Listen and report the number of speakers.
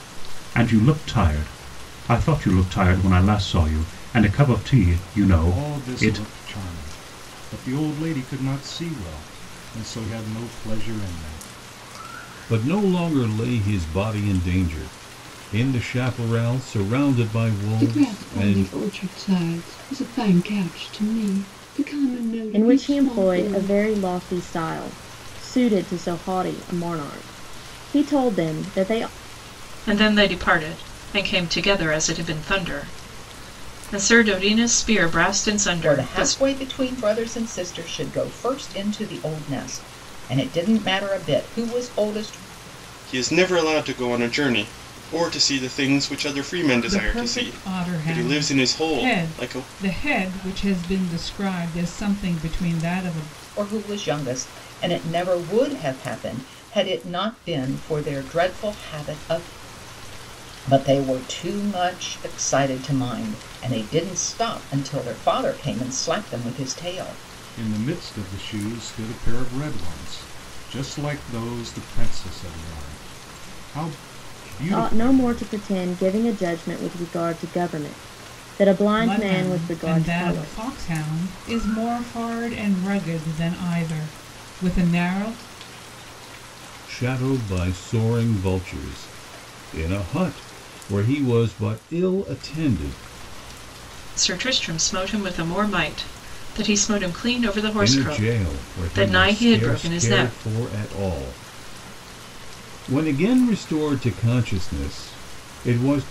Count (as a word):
nine